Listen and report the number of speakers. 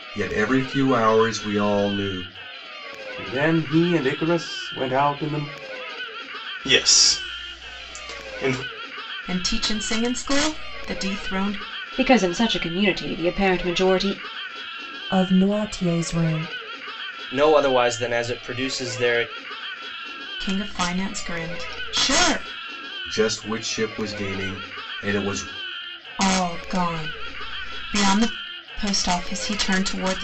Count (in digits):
7